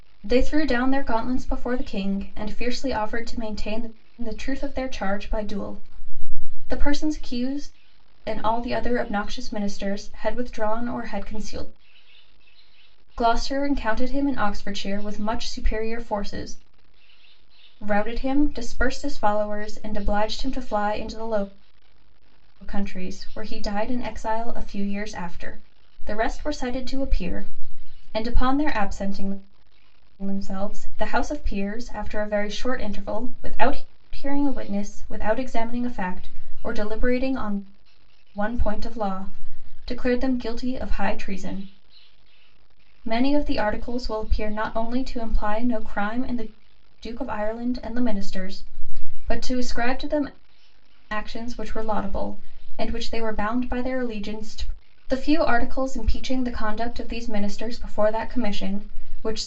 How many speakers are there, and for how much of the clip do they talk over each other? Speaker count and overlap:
1, no overlap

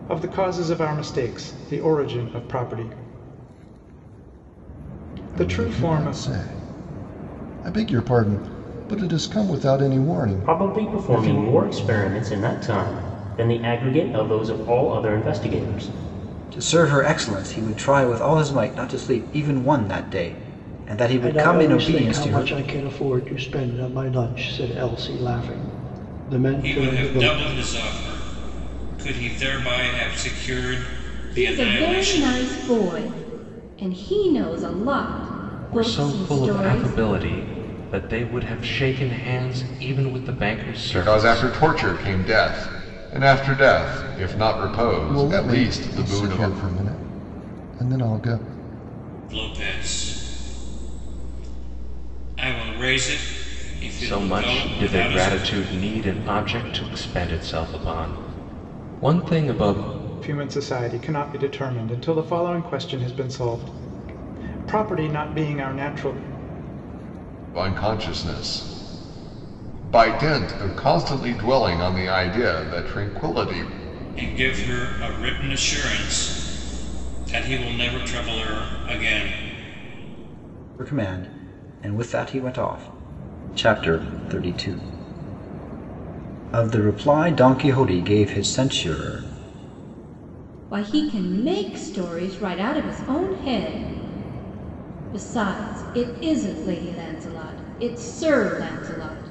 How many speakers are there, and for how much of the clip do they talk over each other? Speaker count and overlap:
9, about 10%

